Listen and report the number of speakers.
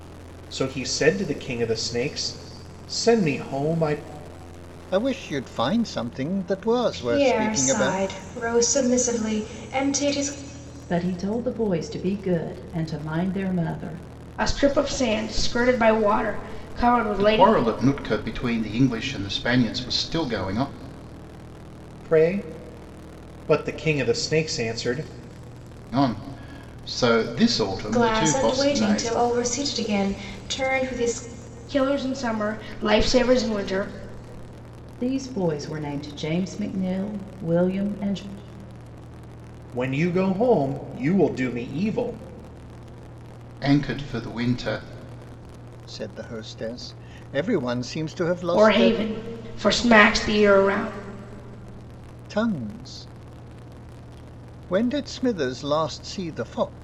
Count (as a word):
six